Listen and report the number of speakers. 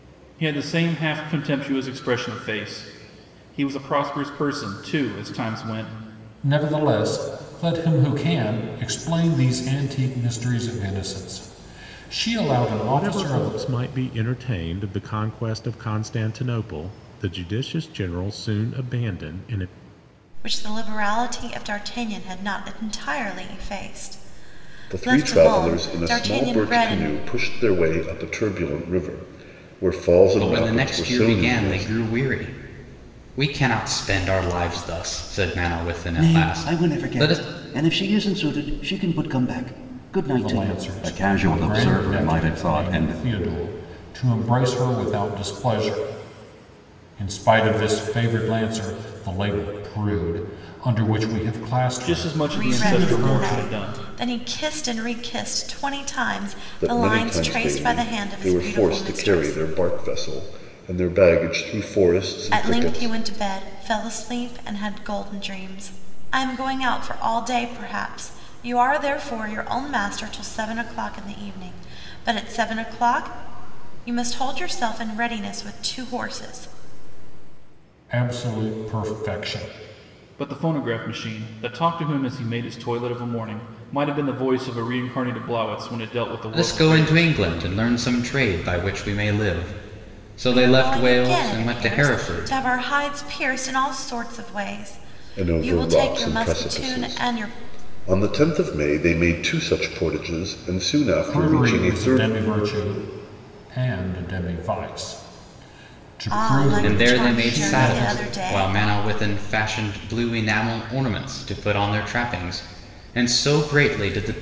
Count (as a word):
seven